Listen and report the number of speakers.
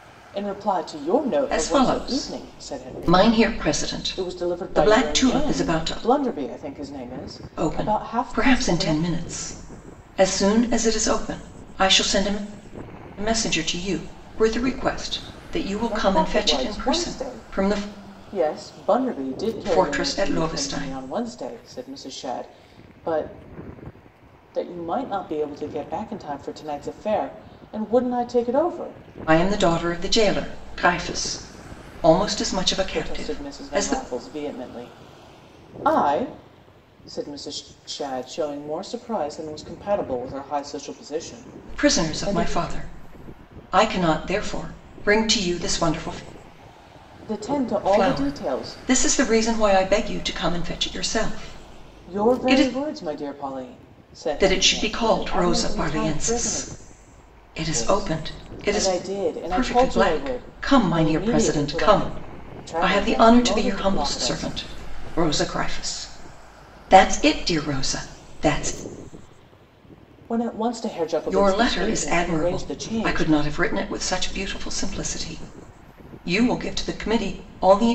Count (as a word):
two